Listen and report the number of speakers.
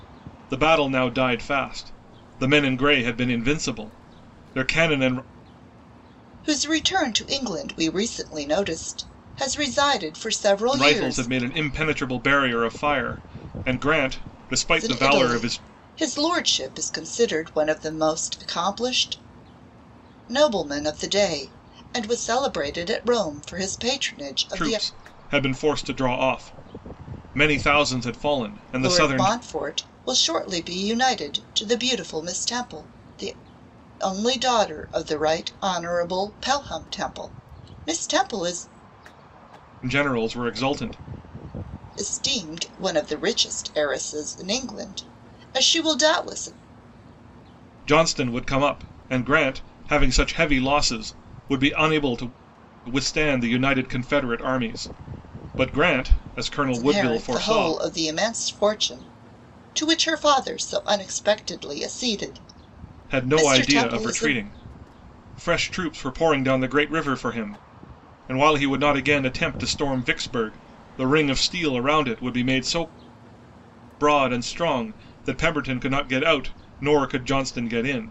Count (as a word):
two